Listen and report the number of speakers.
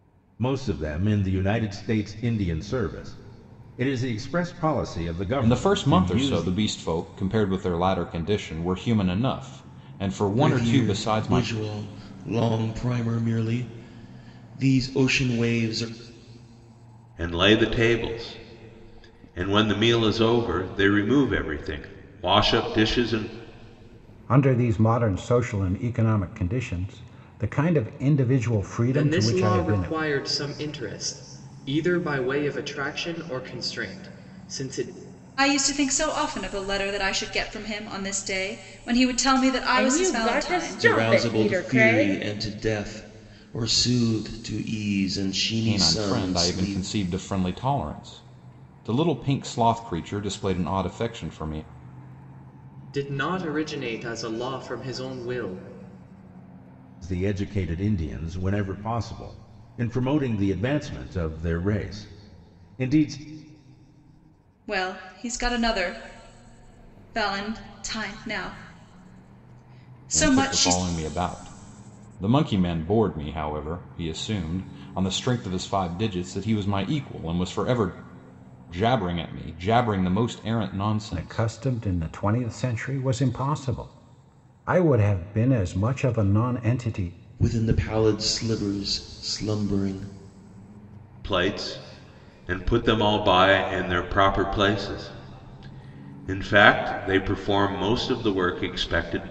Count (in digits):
8